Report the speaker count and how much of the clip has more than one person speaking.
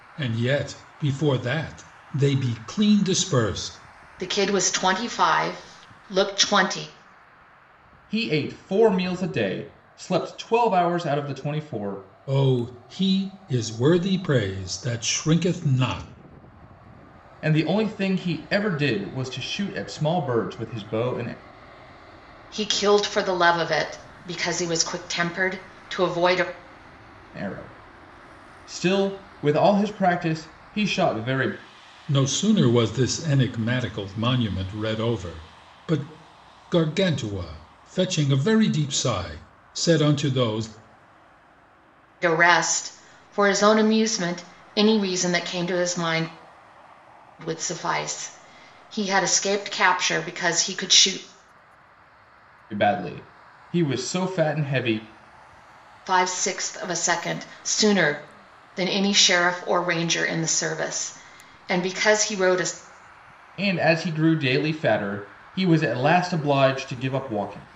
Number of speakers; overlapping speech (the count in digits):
3, no overlap